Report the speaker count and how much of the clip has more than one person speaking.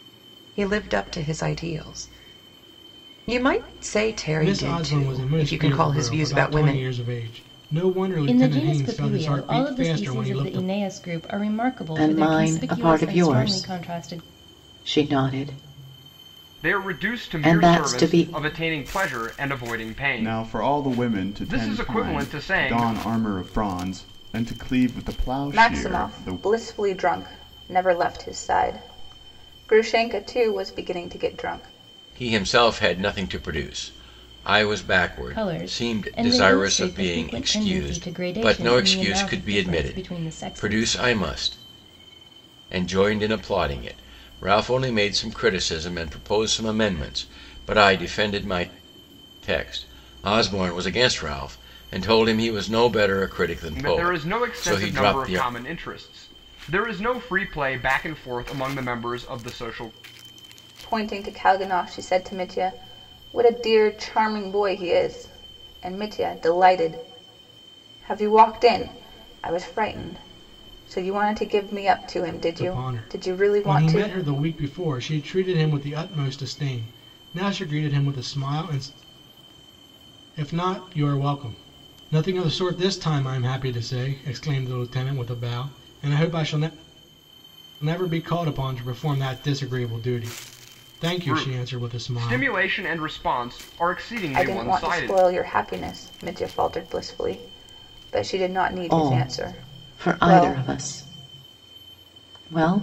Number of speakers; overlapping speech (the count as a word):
eight, about 25%